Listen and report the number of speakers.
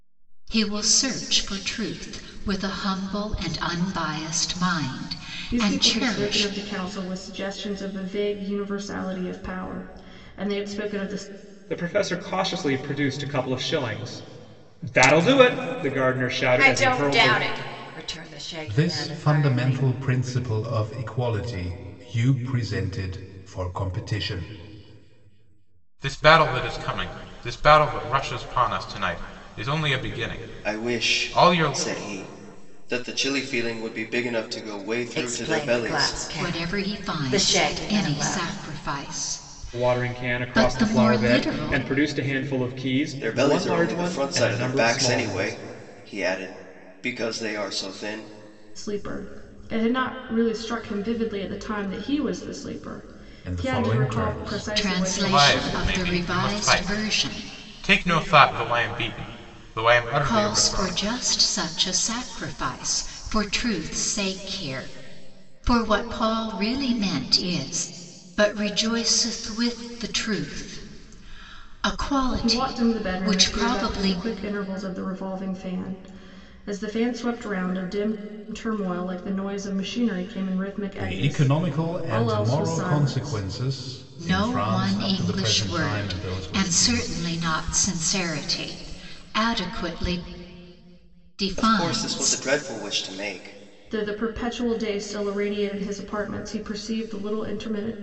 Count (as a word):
seven